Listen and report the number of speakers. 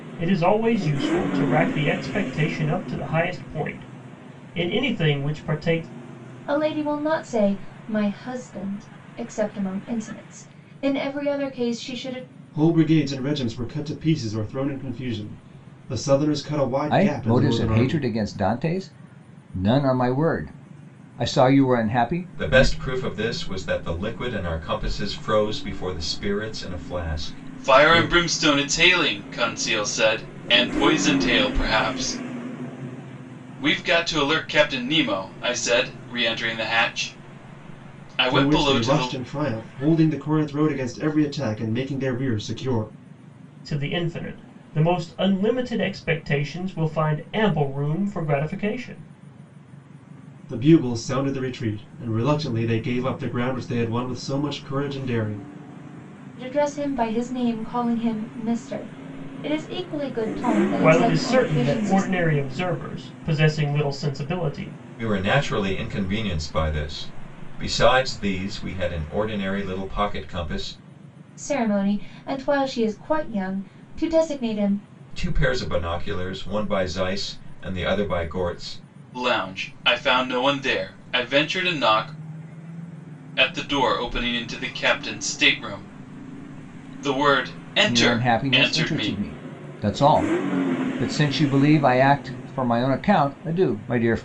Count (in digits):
6